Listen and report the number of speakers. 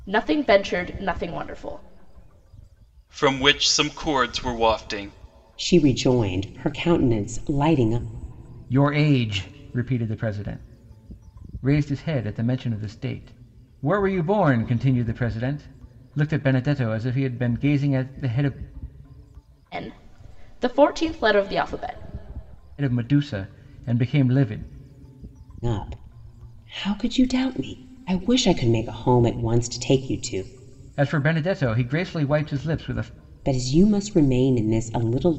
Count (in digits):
4